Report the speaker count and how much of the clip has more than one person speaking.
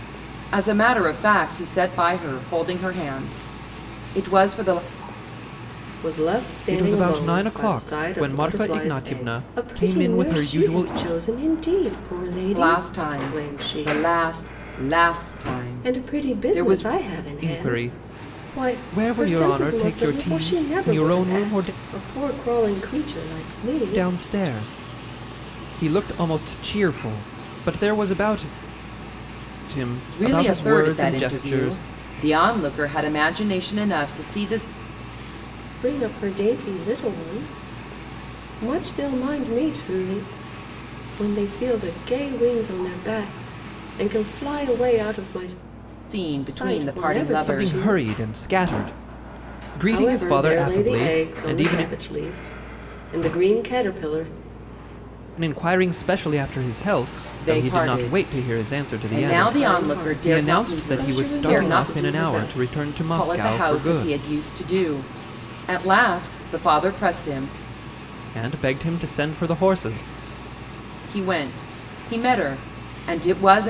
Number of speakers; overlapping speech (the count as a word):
three, about 32%